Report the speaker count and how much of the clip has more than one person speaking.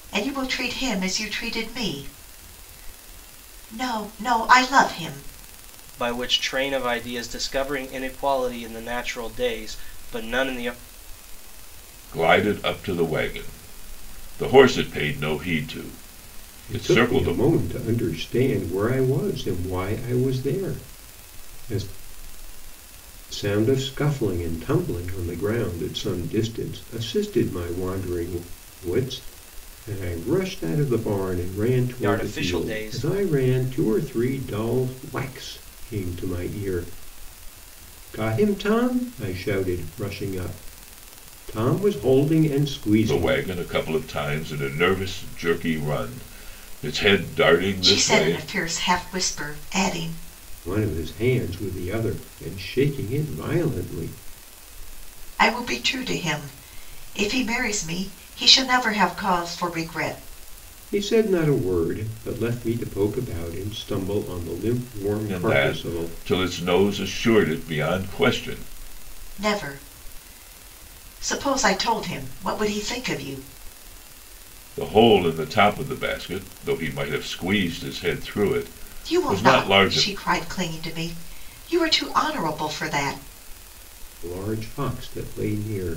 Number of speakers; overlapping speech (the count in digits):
4, about 5%